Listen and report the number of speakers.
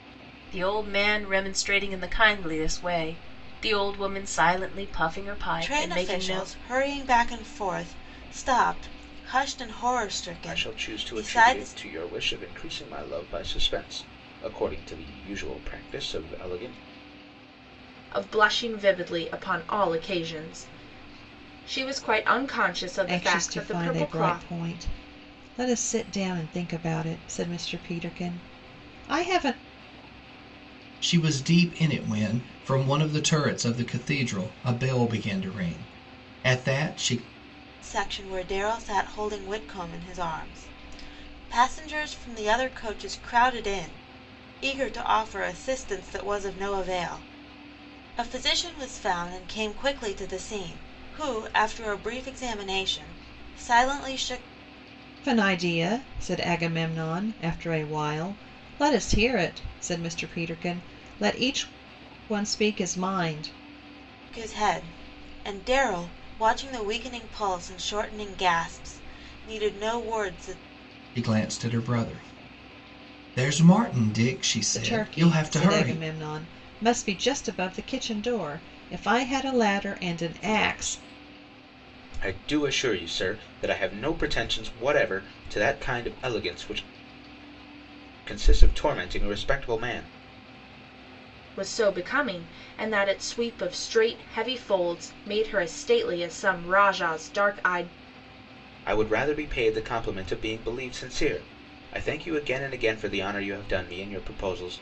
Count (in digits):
6